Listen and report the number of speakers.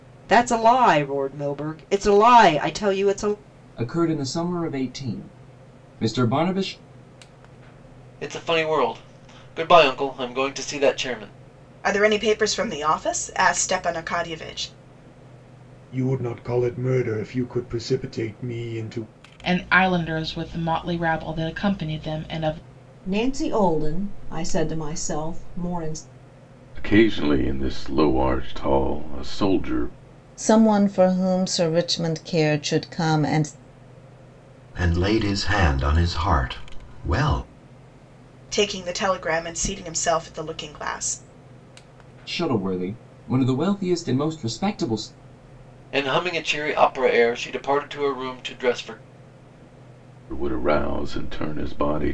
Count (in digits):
10